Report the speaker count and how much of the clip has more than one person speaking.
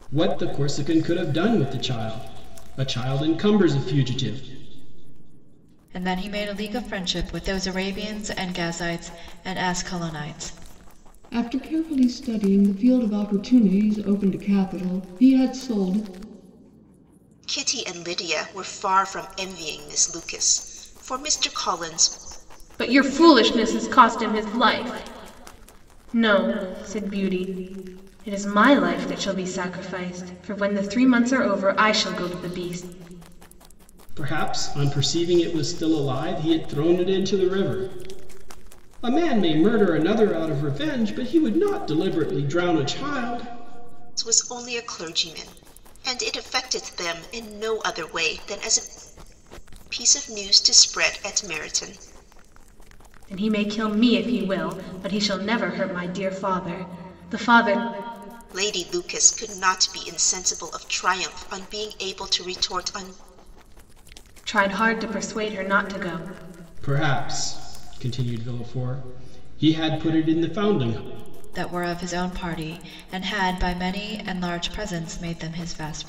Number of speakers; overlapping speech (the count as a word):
five, no overlap